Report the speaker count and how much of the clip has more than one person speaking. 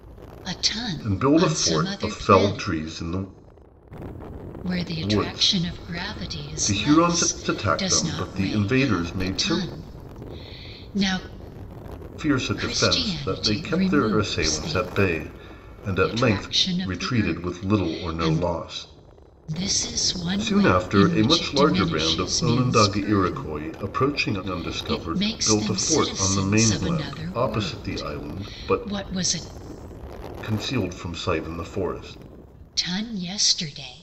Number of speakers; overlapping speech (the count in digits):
2, about 57%